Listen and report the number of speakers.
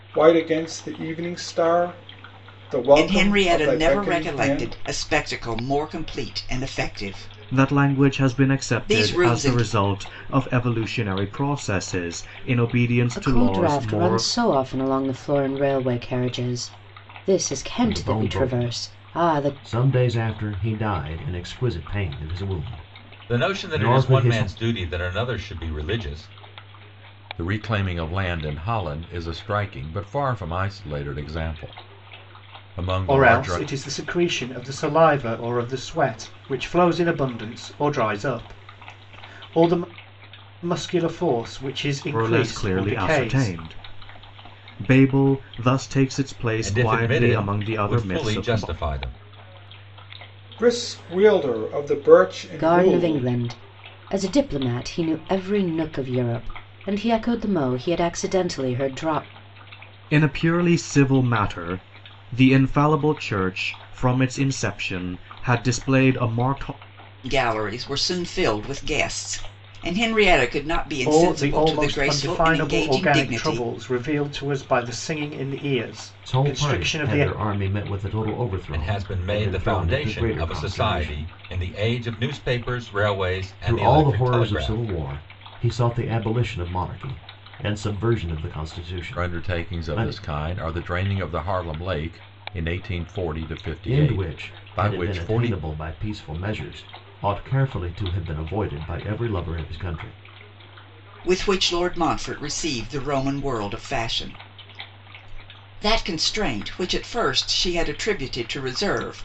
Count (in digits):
8